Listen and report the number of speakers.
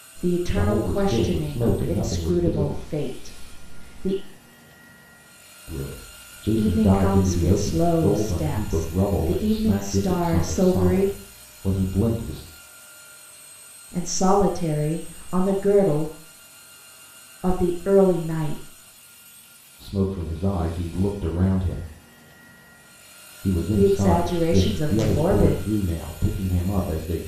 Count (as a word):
two